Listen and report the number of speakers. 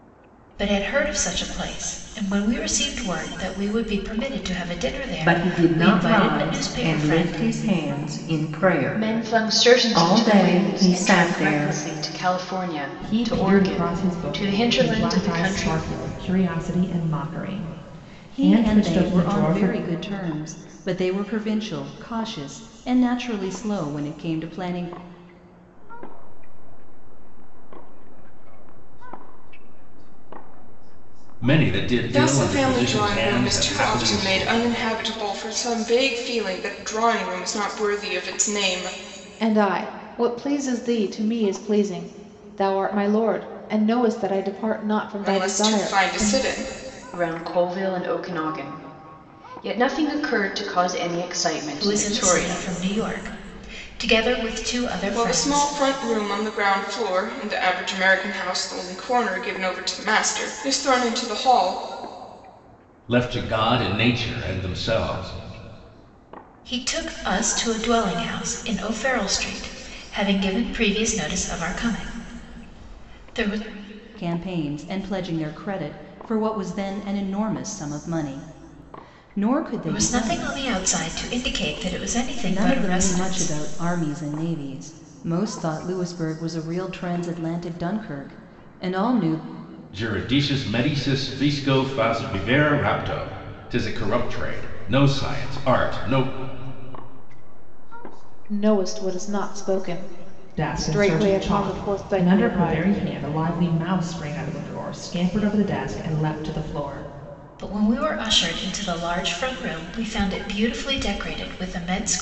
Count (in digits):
9